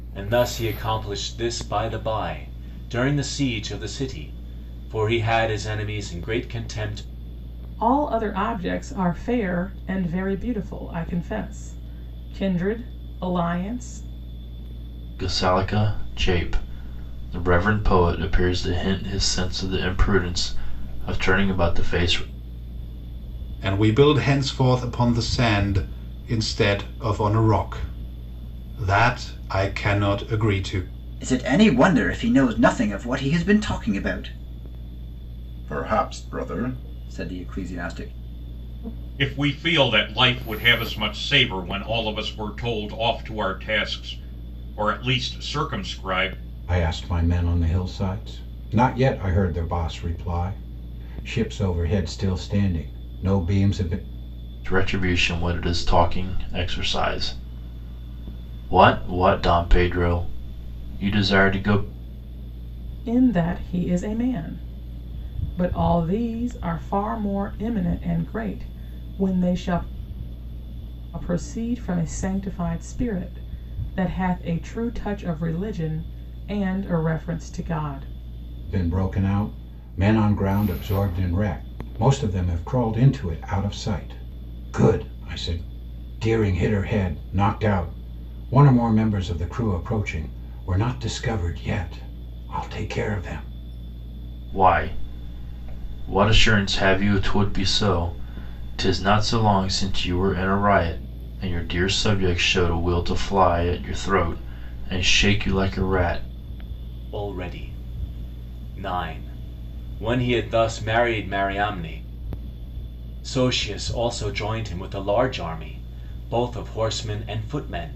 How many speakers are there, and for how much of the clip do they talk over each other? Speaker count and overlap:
seven, no overlap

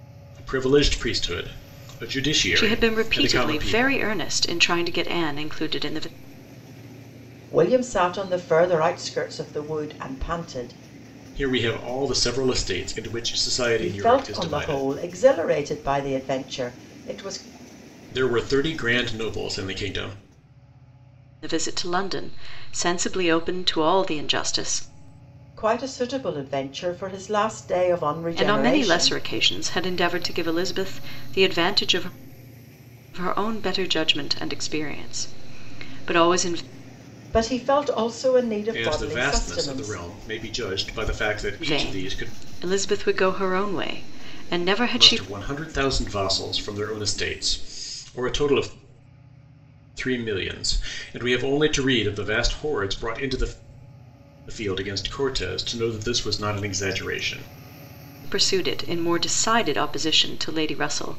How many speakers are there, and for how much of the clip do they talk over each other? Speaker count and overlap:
three, about 10%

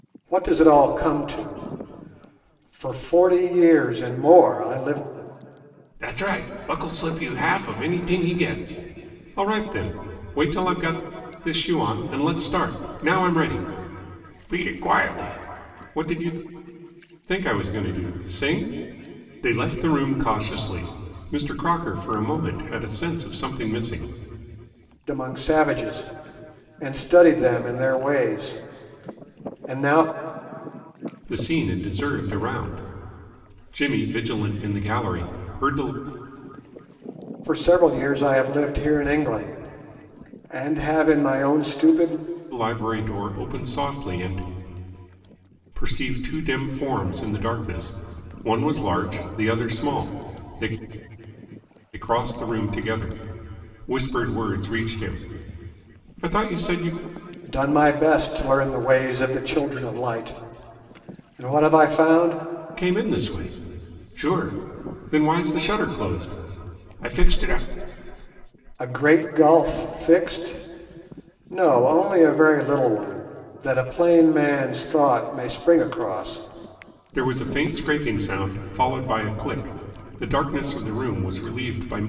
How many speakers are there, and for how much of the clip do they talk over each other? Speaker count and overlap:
two, no overlap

